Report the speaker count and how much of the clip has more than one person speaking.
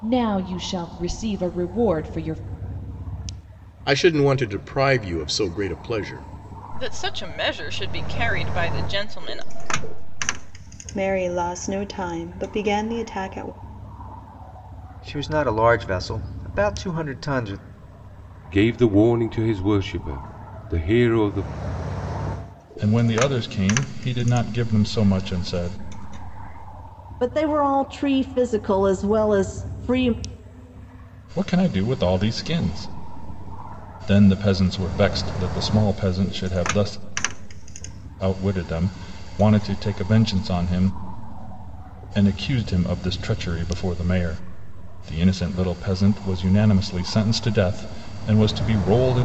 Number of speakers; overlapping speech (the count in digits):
8, no overlap